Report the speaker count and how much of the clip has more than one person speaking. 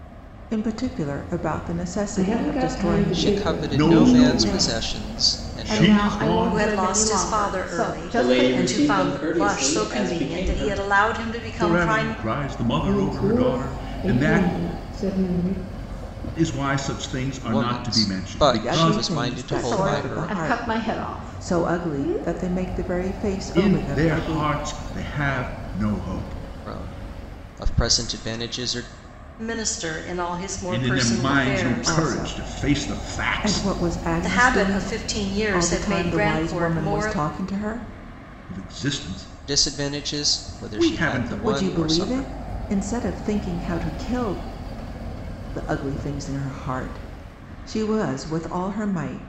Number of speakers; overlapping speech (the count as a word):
seven, about 49%